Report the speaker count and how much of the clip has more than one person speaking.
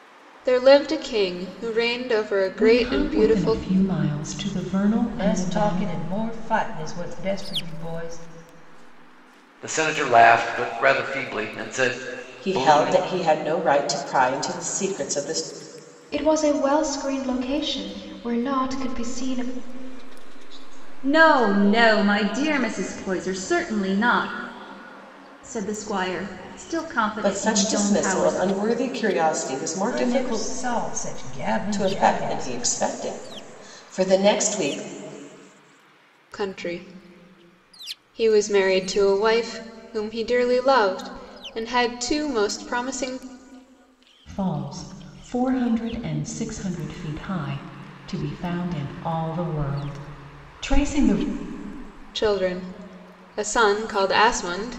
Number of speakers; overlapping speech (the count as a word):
eight, about 14%